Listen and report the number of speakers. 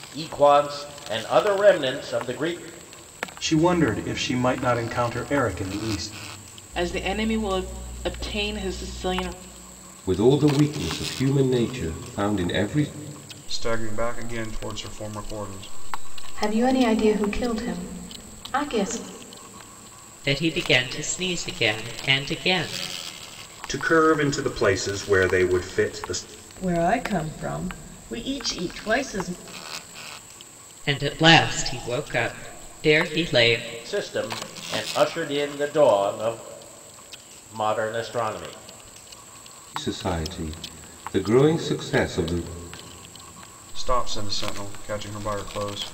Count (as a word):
nine